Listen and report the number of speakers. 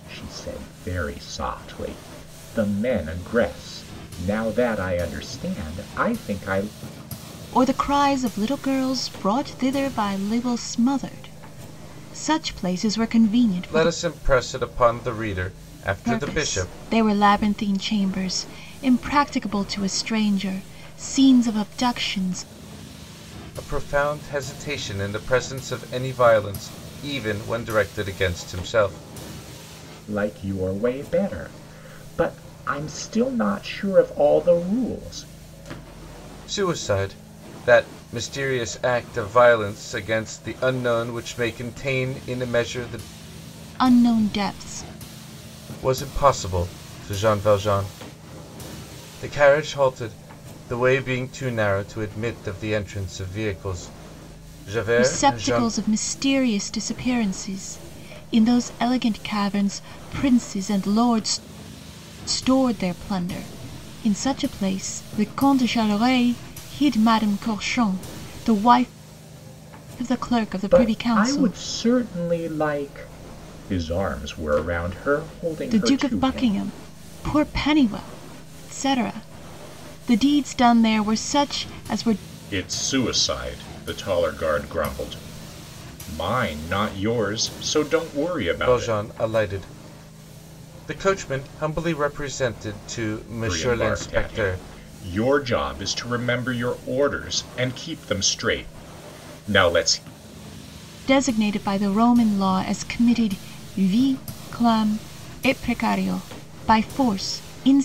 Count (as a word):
three